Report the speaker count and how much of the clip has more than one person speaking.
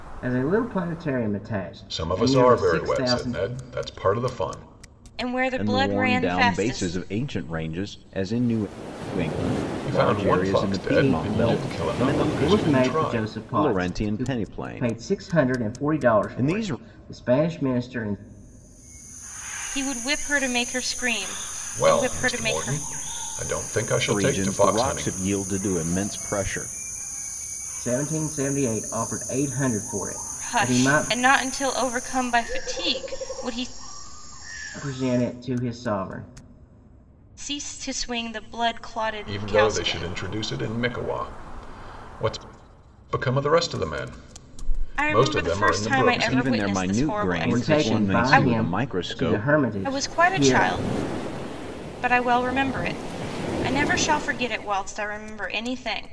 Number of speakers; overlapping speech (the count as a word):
four, about 33%